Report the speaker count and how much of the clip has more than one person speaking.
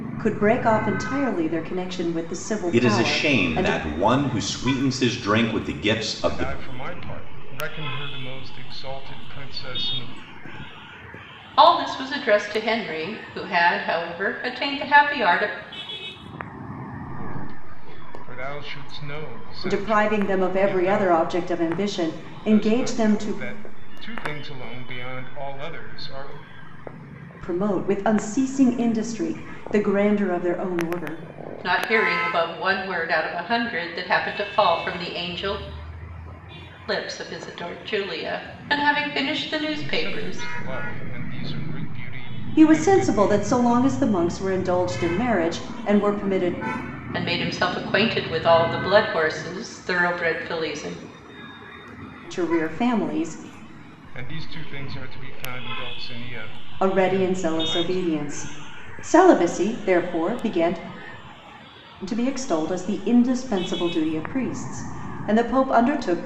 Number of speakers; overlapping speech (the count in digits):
4, about 11%